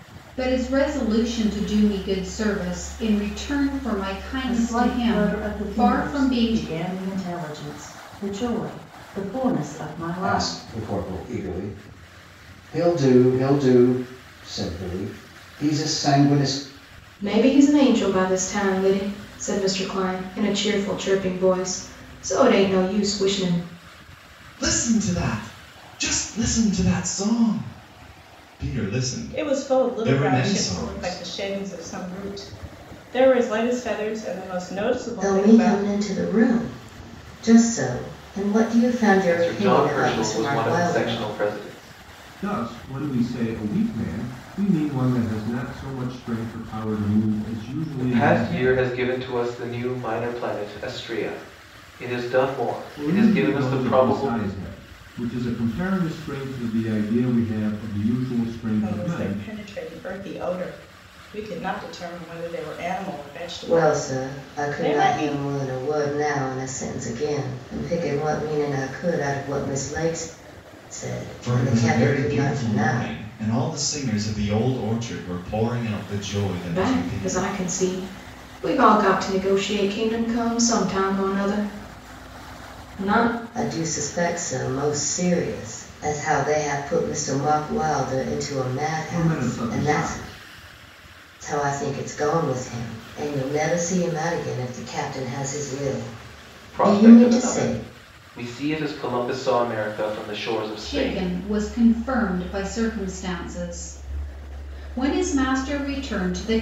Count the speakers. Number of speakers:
9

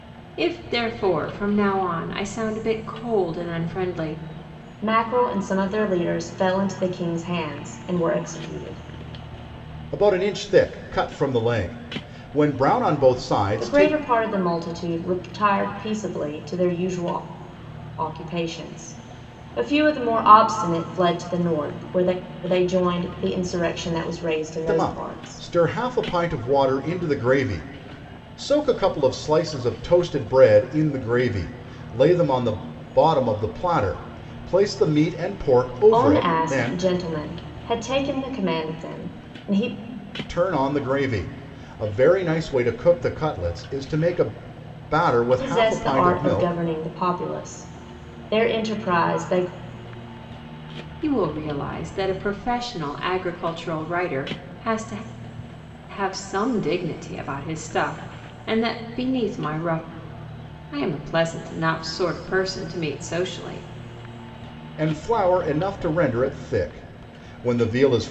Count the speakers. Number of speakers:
3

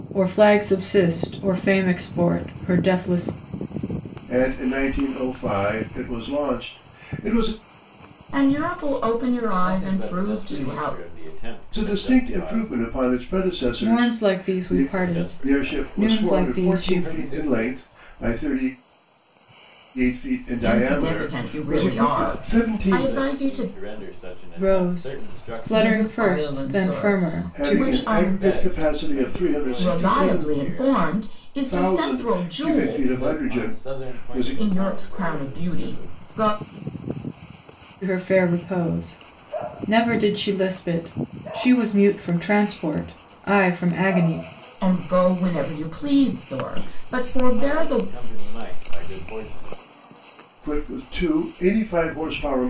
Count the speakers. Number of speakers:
4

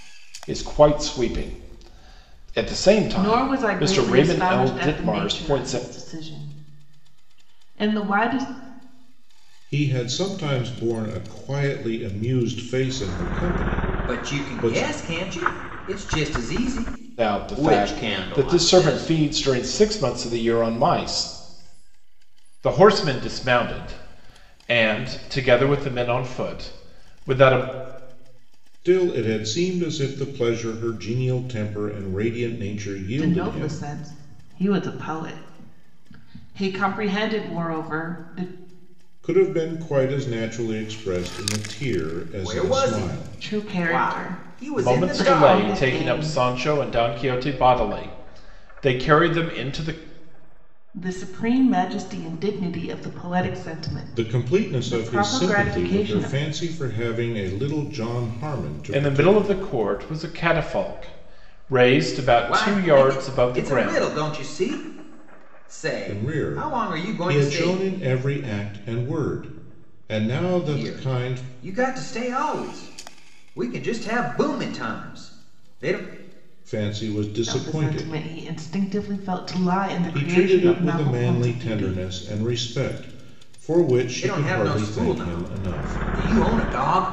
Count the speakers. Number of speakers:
4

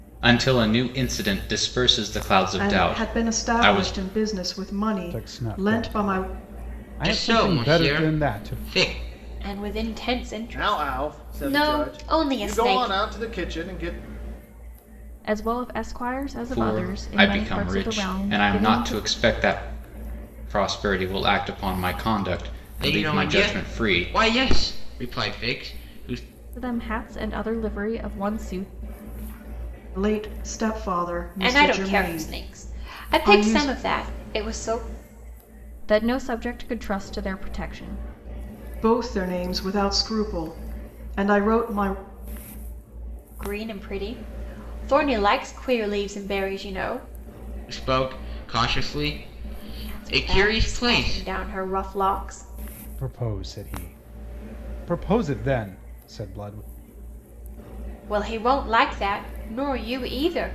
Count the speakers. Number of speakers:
7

